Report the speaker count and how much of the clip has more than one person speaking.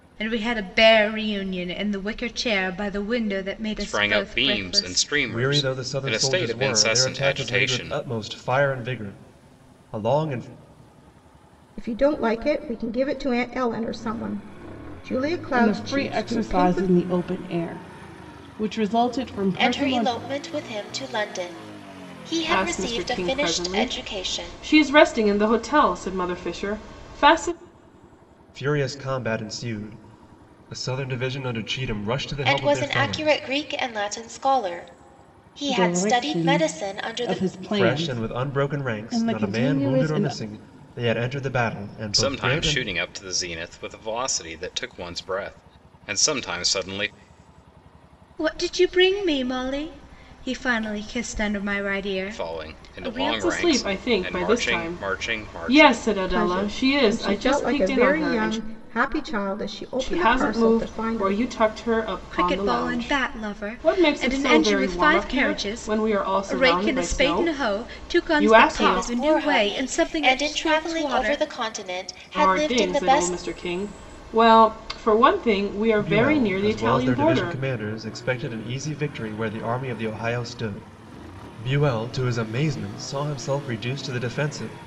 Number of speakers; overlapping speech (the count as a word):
seven, about 39%